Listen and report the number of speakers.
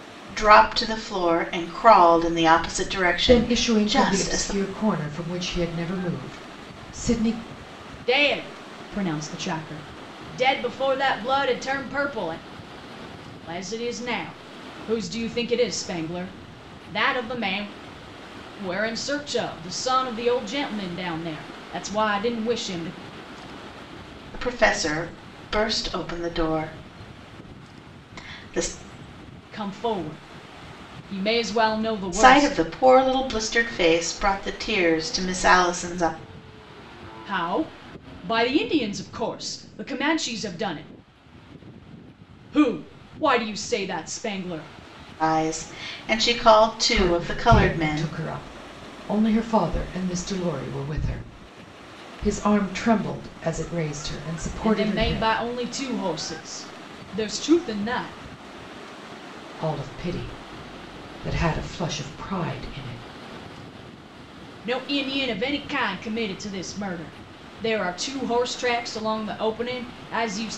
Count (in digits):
3